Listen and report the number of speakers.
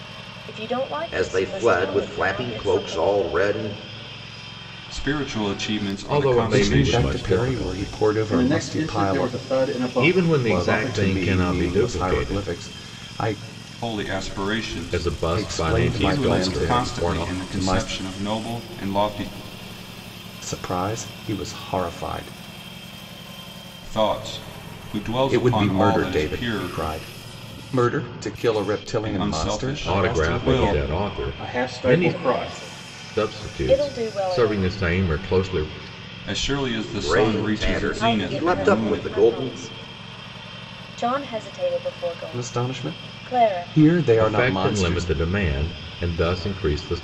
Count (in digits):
6